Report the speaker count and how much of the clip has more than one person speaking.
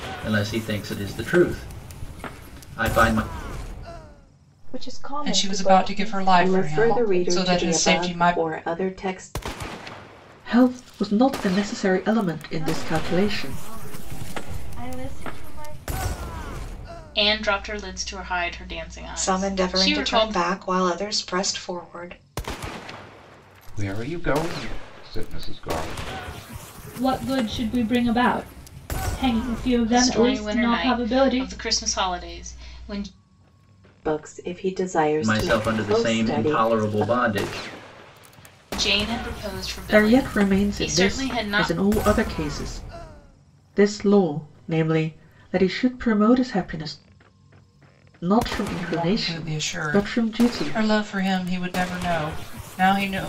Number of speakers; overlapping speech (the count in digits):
10, about 25%